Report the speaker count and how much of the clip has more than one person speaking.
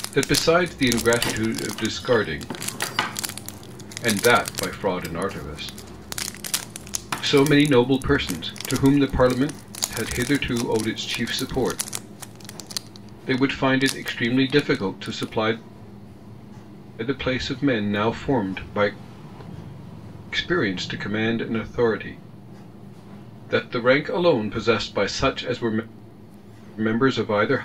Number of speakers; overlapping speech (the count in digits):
1, no overlap